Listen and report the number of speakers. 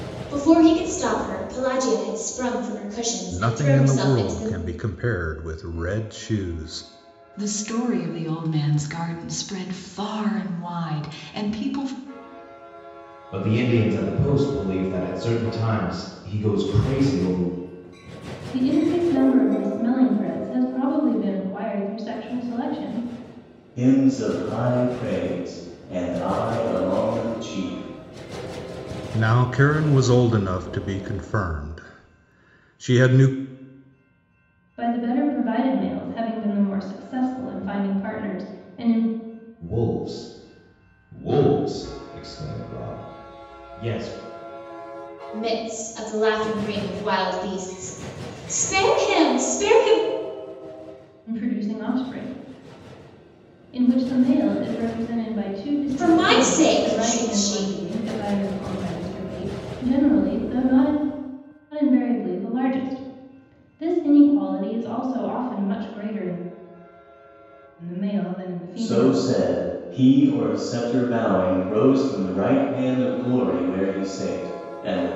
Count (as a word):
six